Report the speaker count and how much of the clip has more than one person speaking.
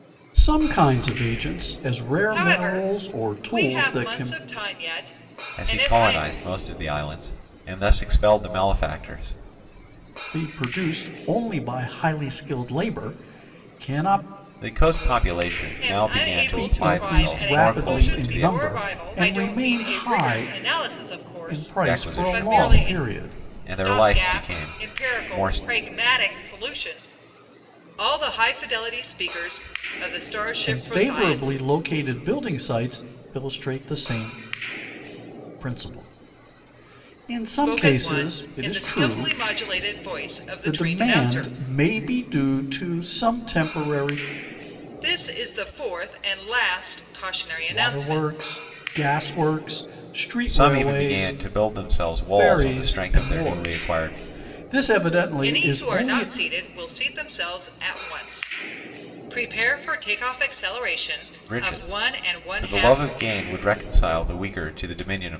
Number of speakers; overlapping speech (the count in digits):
3, about 32%